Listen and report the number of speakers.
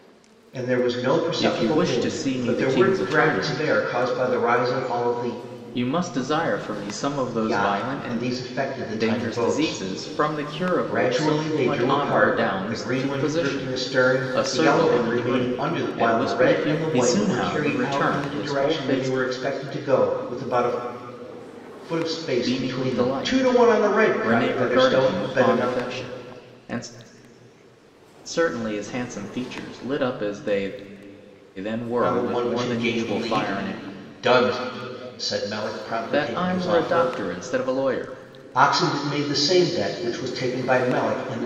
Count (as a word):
two